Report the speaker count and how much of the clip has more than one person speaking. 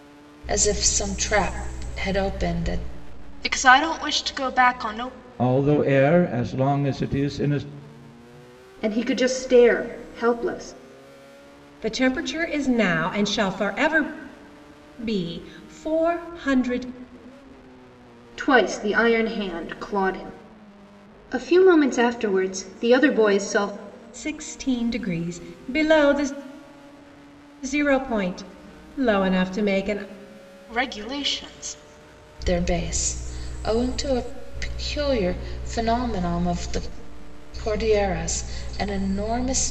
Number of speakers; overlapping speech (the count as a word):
five, no overlap